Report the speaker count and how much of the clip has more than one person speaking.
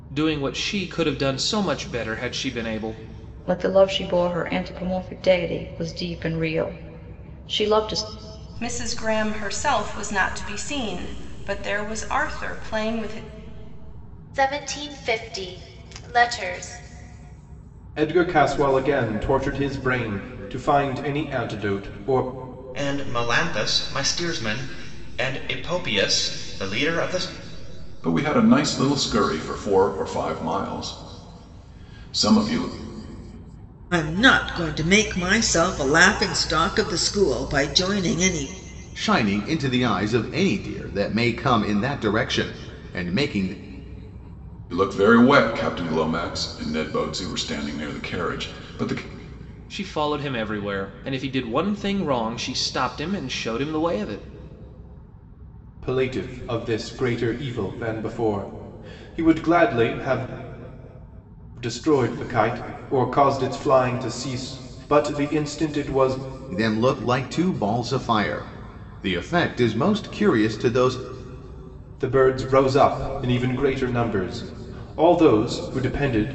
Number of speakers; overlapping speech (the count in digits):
9, no overlap